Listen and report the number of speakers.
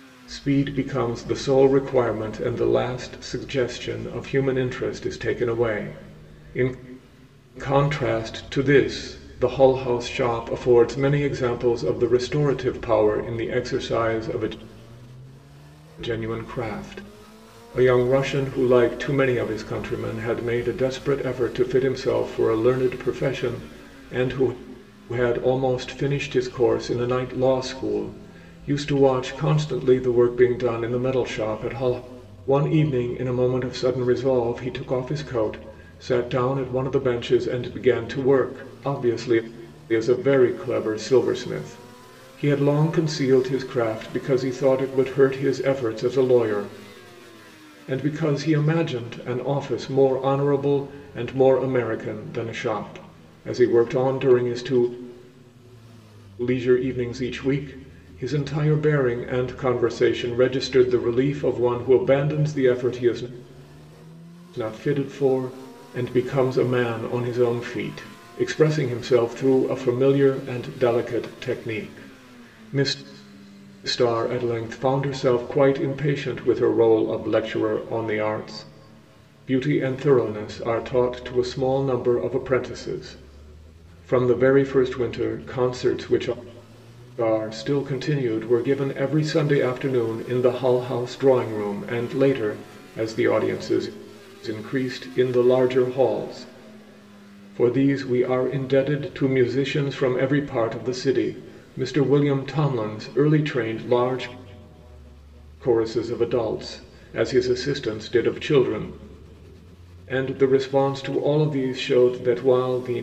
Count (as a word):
one